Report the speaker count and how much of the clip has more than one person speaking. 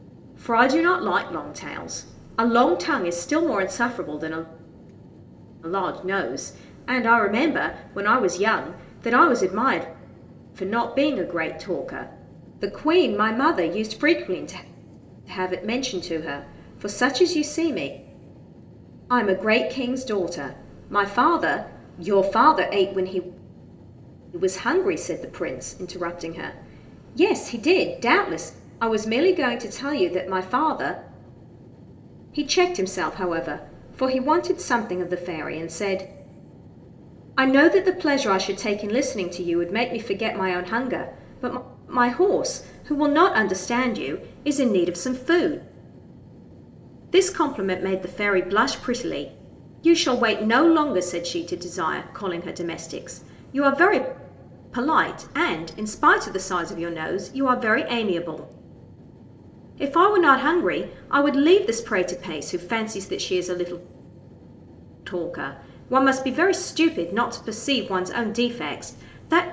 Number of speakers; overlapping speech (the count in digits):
1, no overlap